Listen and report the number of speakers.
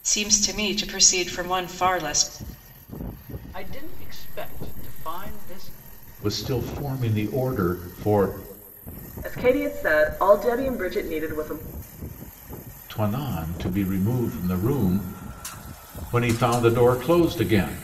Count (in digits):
4